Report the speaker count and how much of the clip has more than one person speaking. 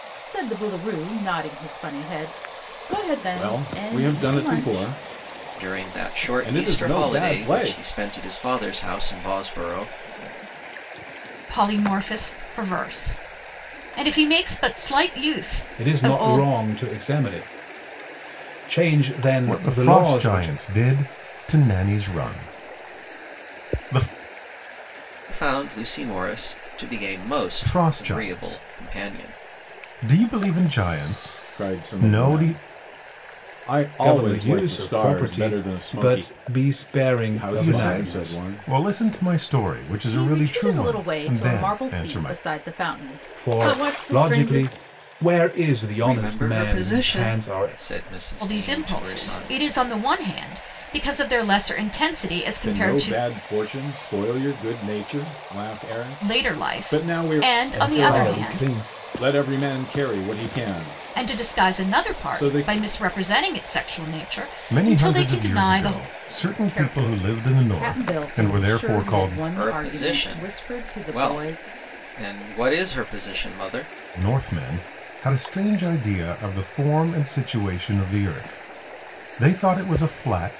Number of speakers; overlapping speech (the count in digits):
6, about 37%